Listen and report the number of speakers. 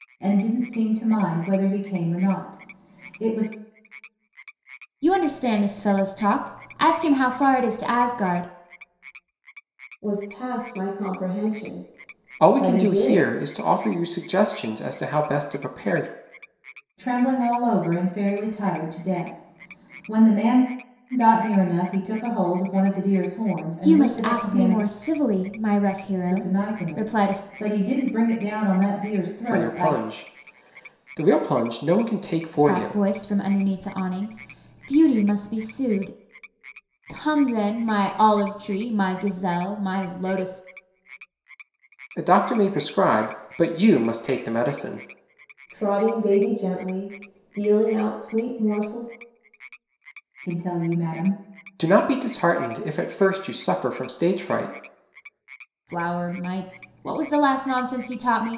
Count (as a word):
four